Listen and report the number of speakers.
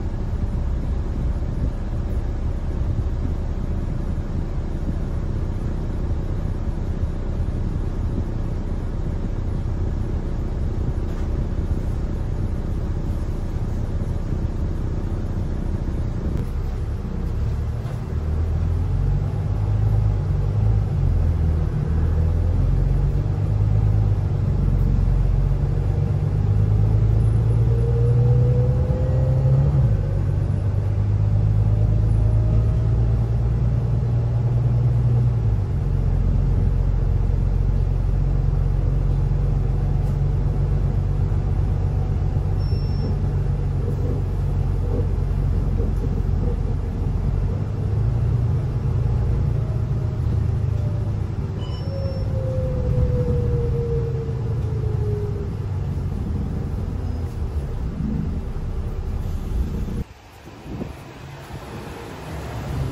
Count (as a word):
zero